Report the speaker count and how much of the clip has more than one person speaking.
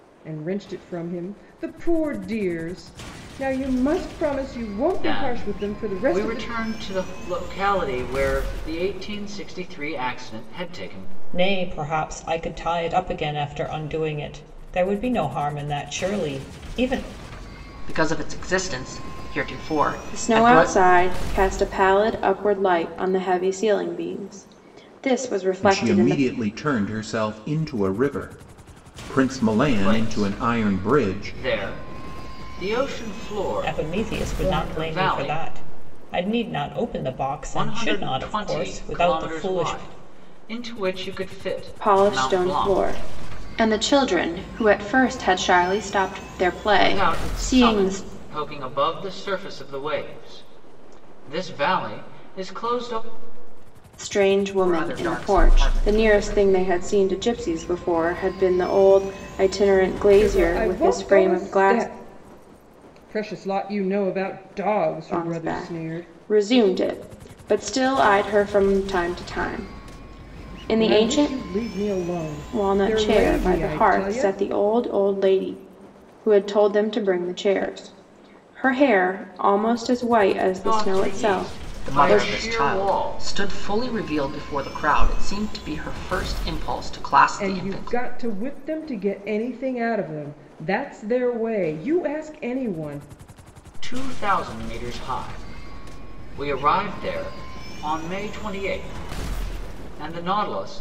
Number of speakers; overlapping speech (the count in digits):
6, about 22%